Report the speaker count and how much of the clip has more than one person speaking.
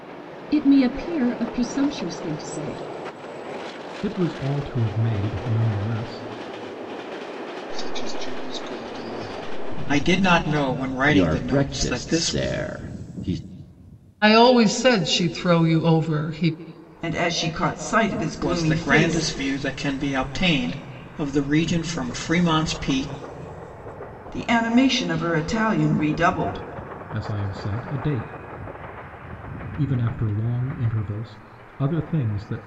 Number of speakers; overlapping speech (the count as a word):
seven, about 7%